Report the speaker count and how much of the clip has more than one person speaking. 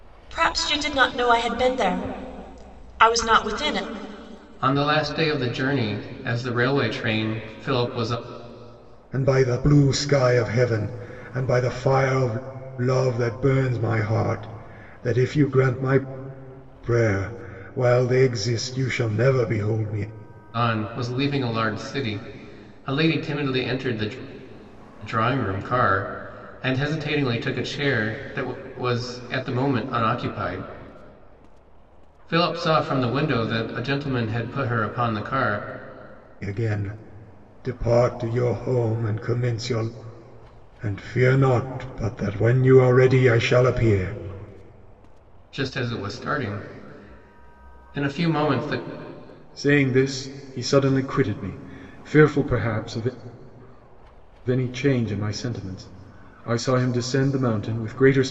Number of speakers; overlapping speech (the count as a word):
three, no overlap